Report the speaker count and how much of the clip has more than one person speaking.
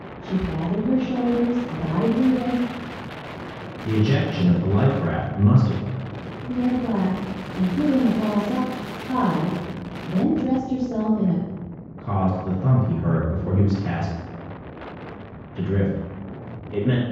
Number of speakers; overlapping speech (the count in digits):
2, no overlap